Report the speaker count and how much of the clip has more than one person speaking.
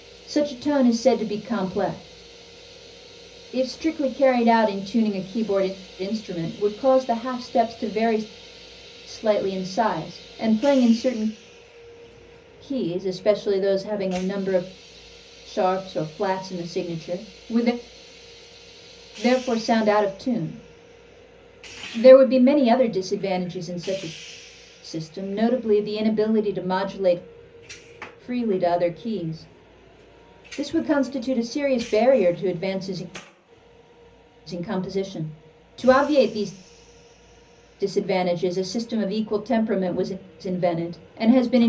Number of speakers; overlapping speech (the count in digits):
1, no overlap